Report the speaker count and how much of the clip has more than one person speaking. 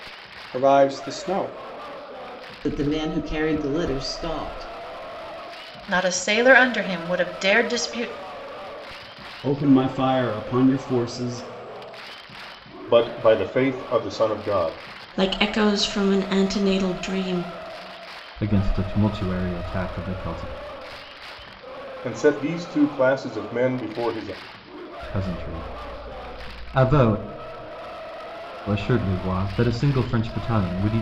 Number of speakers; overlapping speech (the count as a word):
seven, no overlap